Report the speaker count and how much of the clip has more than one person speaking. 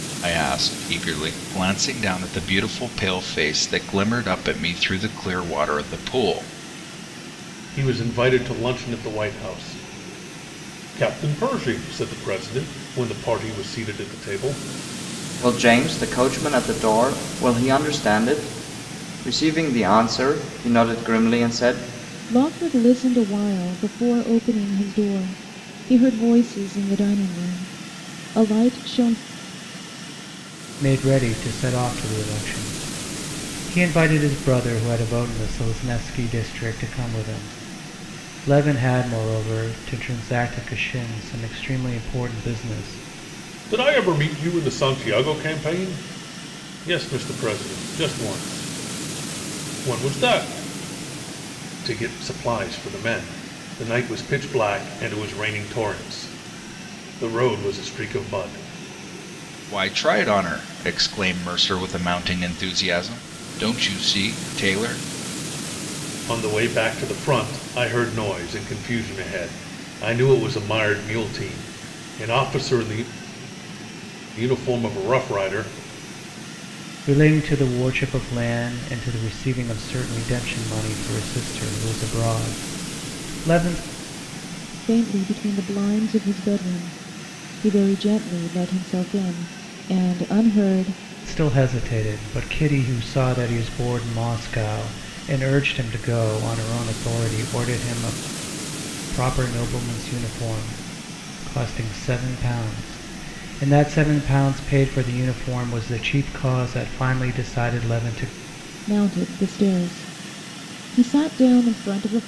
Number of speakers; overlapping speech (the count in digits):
5, no overlap